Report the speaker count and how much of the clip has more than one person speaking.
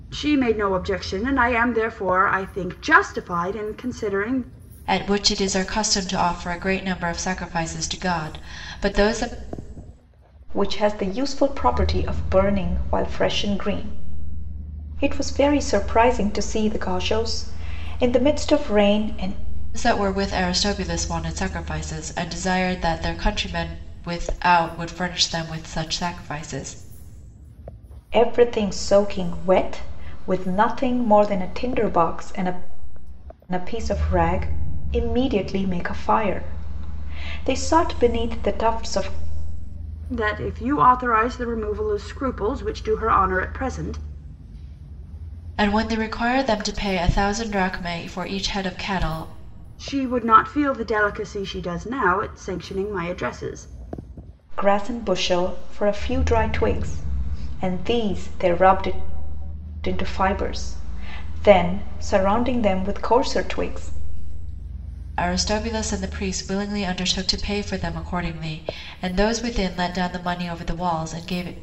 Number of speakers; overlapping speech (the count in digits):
3, no overlap